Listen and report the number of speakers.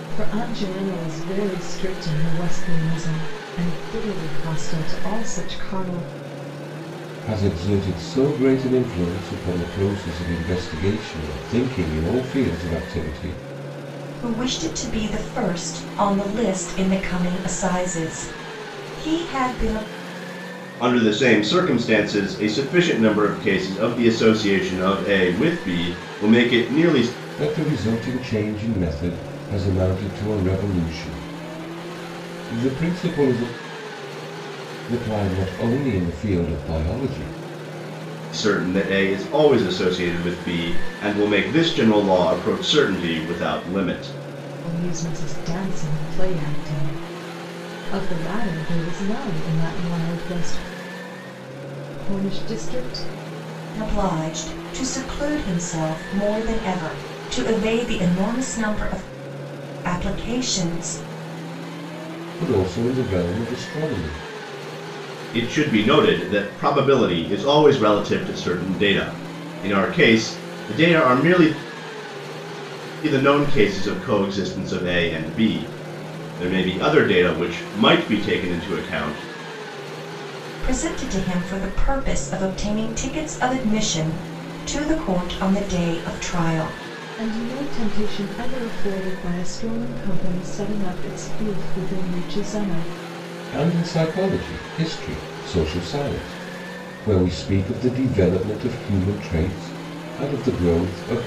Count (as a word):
four